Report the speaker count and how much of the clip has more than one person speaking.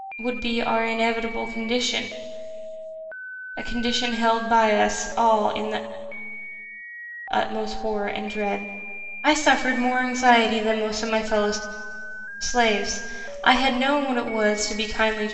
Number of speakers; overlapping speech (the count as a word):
one, no overlap